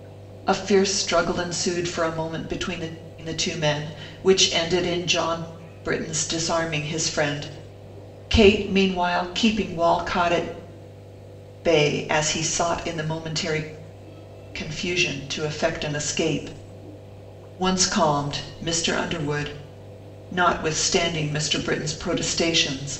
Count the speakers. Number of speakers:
1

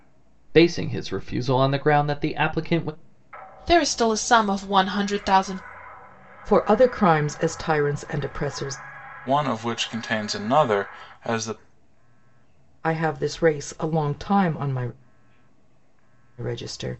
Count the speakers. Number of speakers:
4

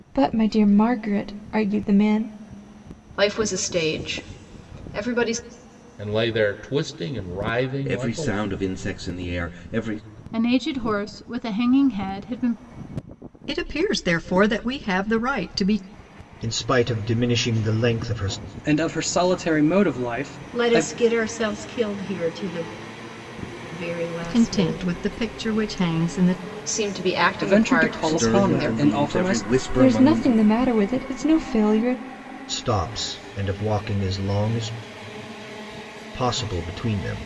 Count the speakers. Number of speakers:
9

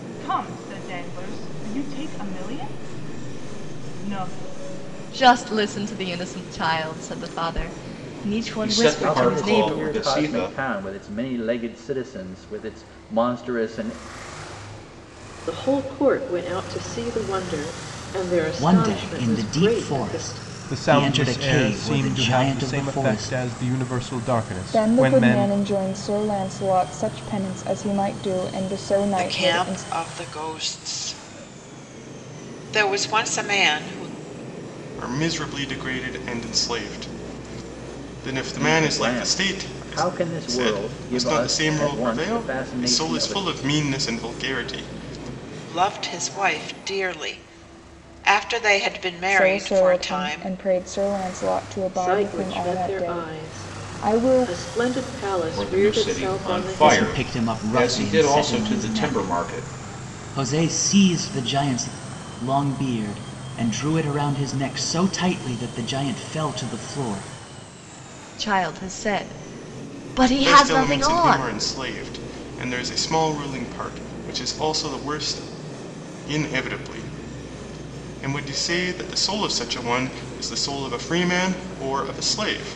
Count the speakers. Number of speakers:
10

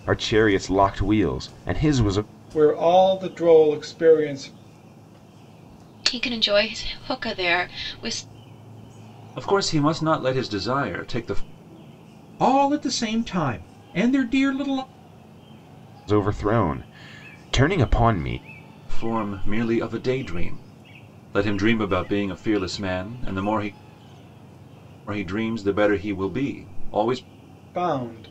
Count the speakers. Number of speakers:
5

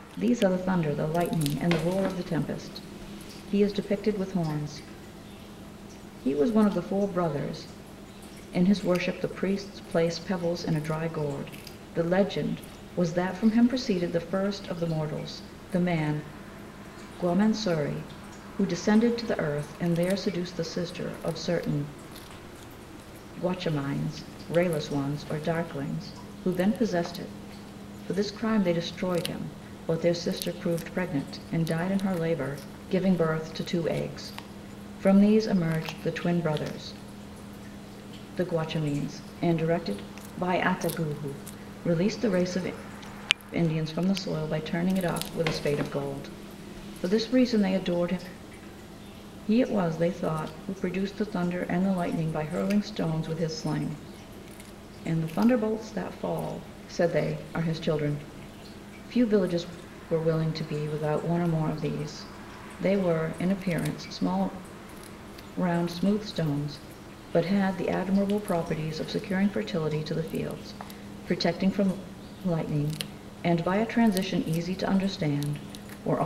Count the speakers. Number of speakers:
1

